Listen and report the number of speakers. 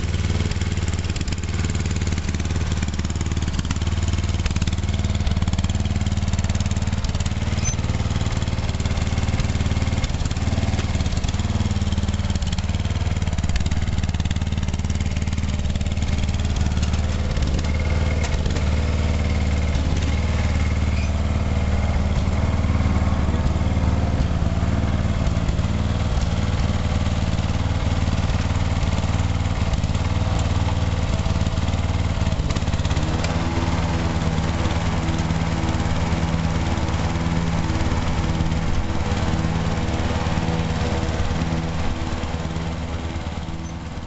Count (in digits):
0